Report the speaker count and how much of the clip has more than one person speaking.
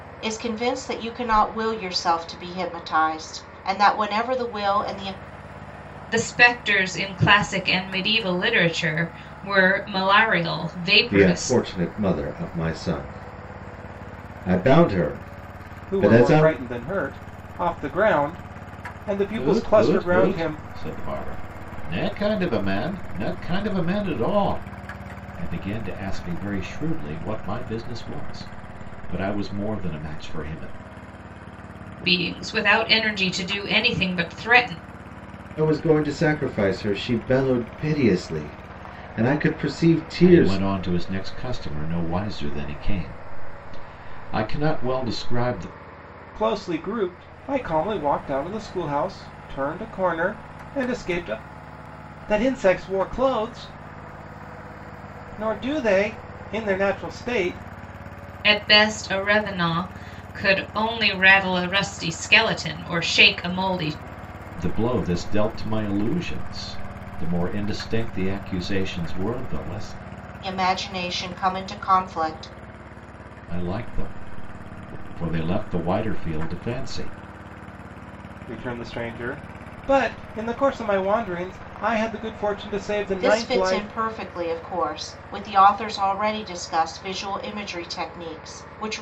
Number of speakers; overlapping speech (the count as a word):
five, about 4%